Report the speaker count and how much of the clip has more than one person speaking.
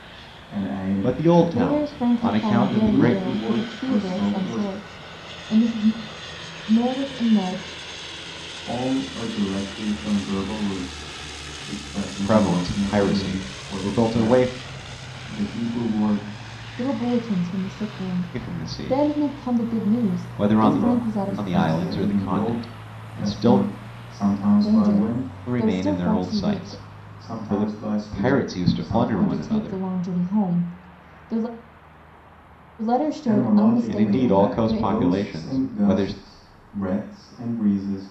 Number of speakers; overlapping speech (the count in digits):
3, about 48%